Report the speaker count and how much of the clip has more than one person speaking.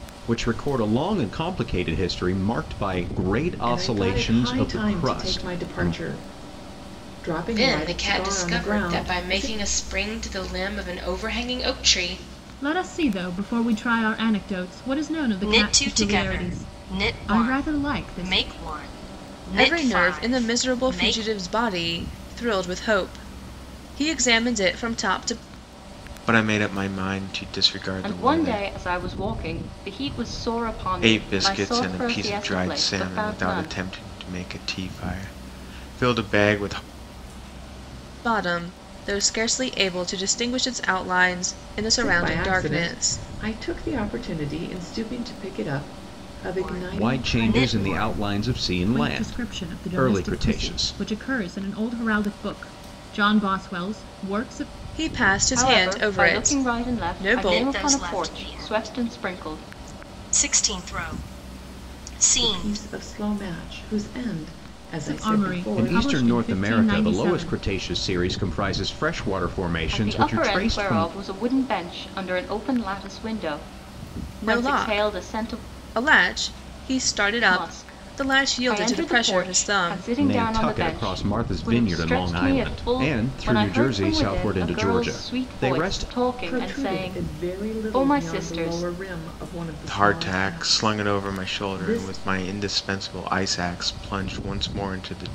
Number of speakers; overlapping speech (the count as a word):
eight, about 43%